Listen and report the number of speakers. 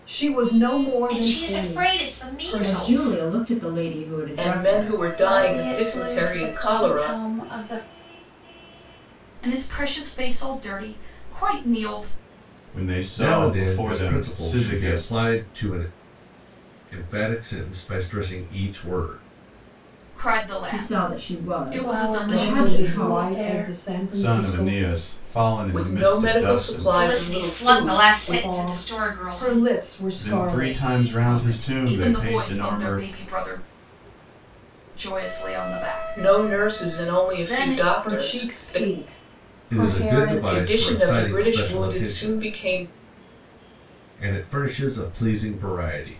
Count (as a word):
eight